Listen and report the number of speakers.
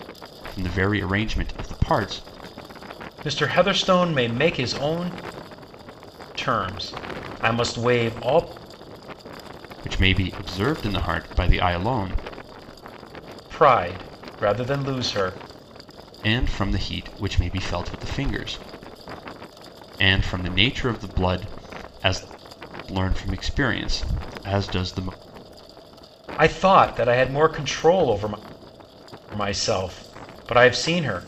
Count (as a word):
two